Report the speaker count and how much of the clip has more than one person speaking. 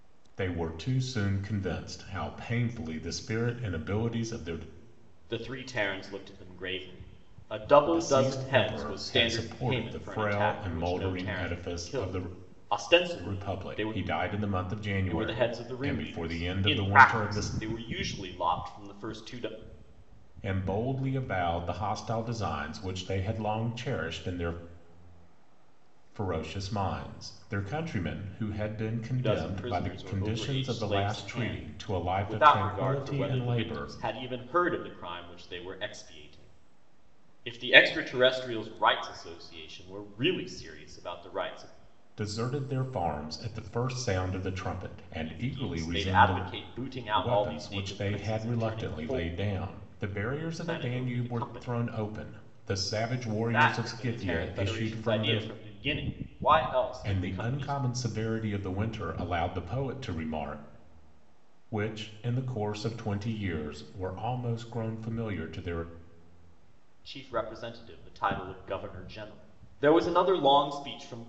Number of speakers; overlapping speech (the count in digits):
2, about 27%